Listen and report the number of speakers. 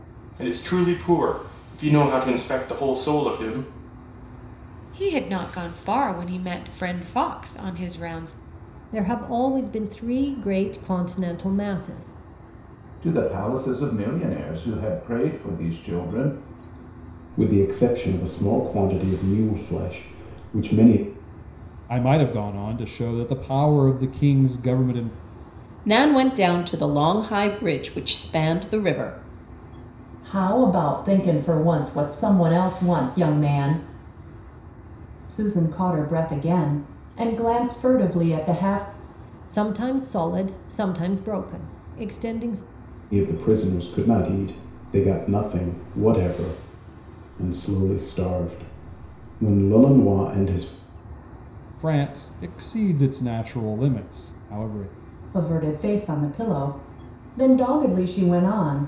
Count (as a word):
eight